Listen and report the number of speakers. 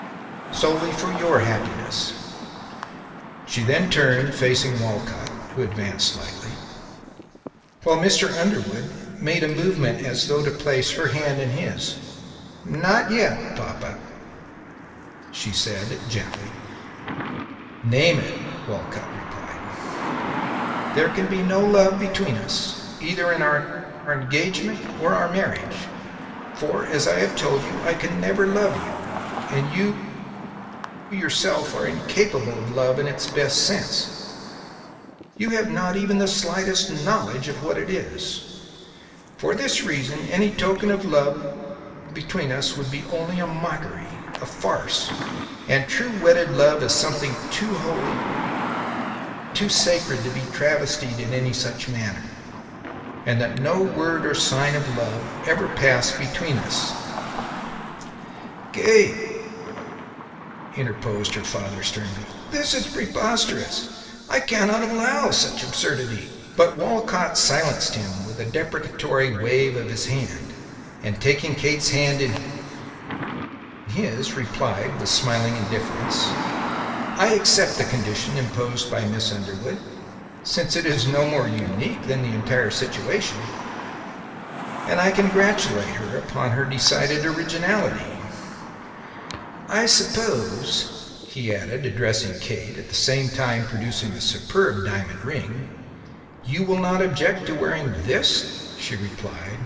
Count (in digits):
1